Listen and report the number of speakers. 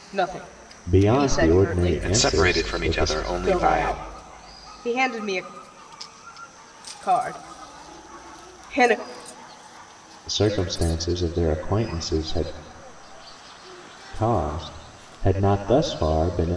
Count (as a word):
three